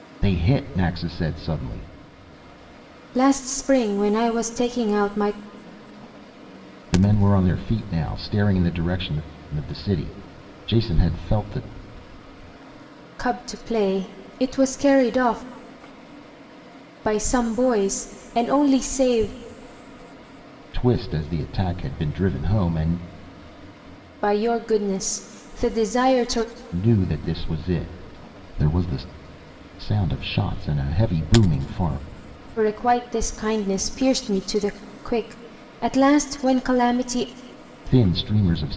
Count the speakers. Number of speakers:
2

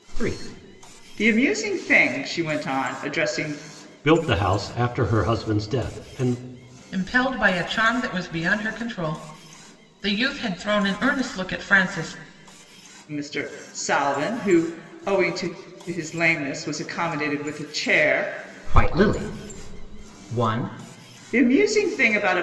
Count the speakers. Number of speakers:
4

